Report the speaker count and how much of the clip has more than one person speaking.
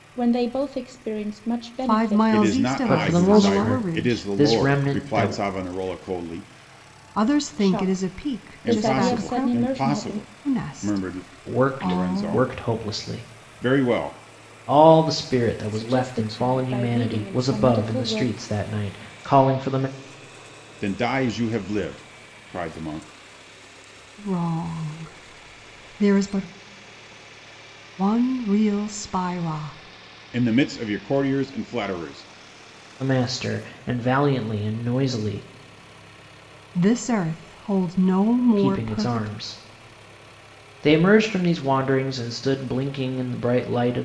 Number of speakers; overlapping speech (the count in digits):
4, about 28%